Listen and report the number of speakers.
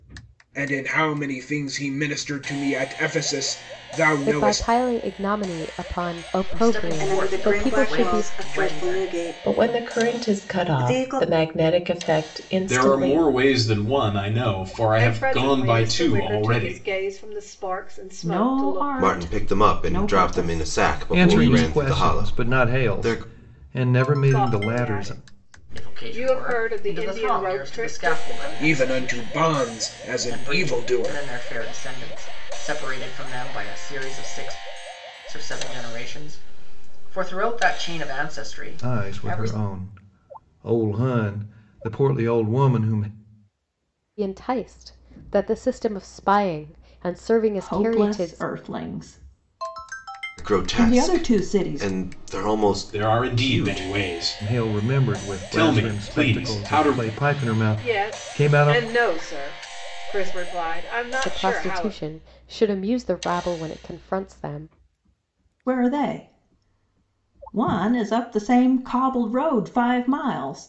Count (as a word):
ten